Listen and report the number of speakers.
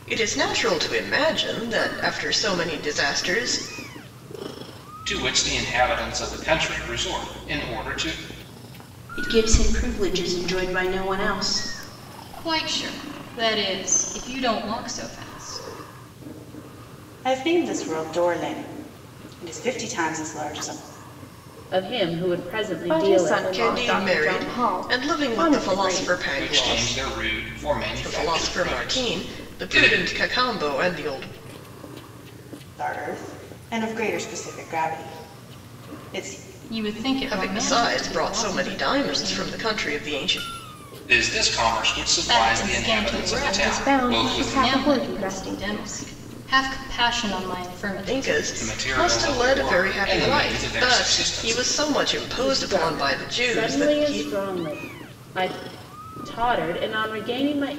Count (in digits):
7